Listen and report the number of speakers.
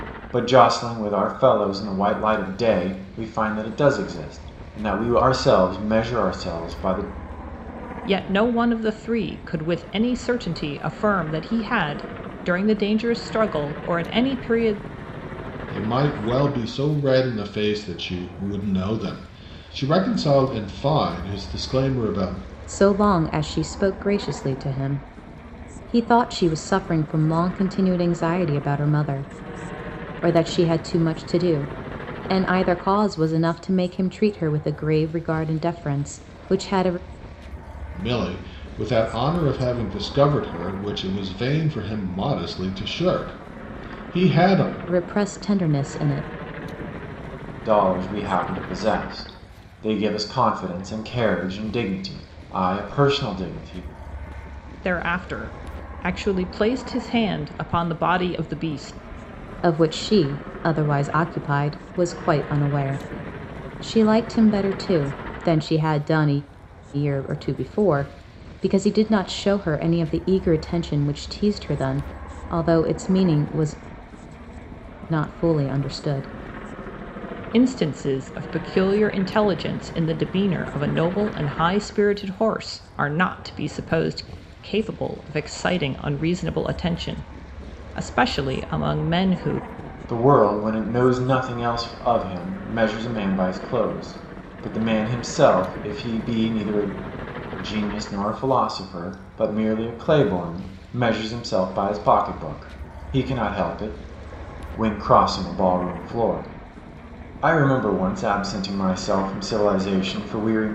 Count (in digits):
4